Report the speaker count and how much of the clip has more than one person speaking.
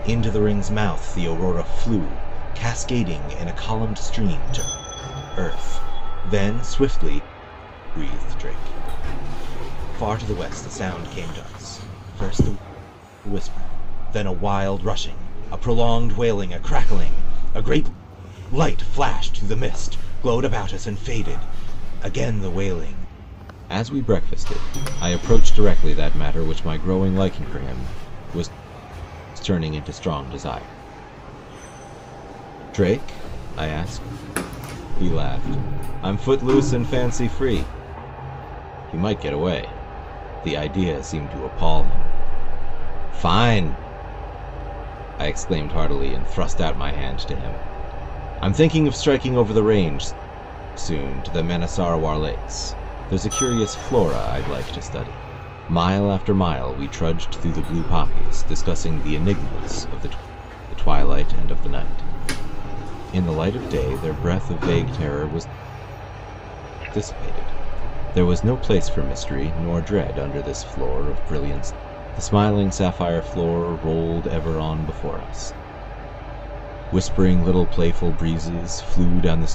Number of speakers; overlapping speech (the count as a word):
one, no overlap